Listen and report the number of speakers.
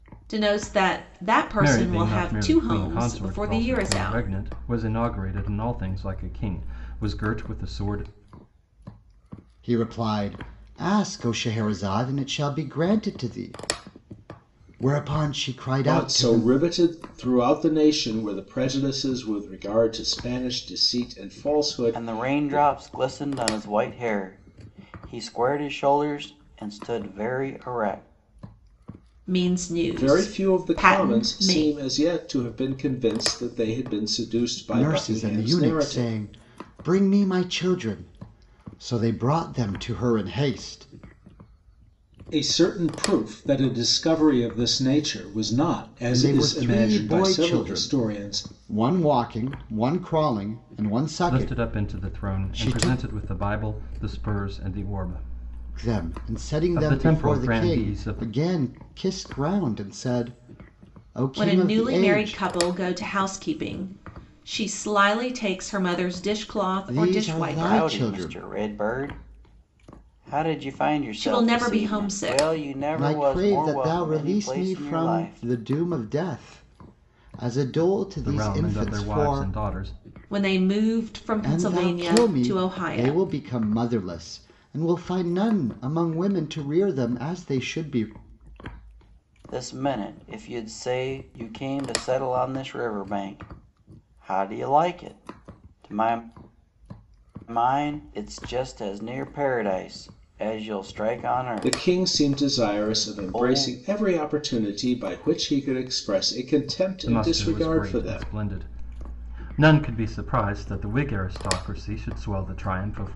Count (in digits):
5